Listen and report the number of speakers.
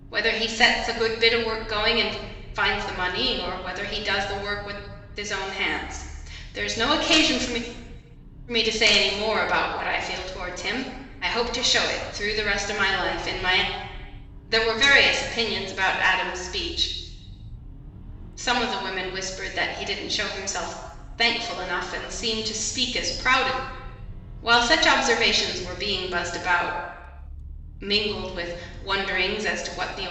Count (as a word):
one